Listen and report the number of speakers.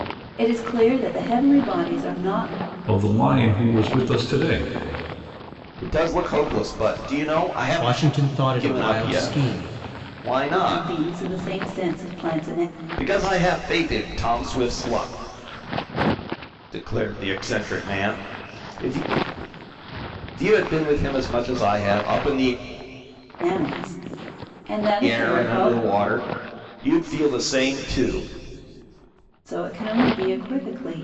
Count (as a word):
four